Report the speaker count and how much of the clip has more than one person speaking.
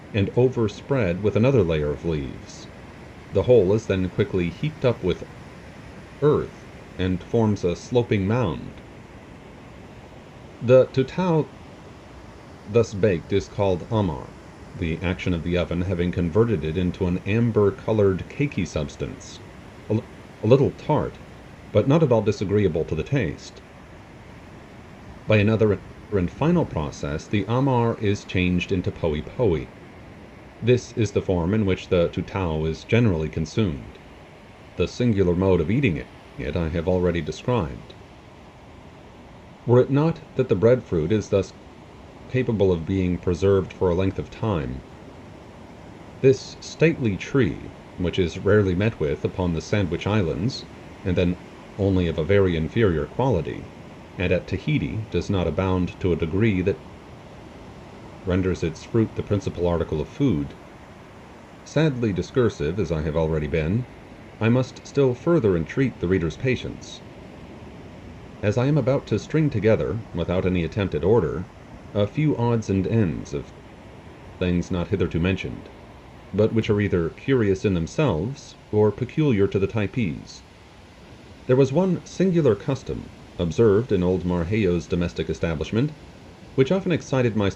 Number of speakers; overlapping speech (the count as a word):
one, no overlap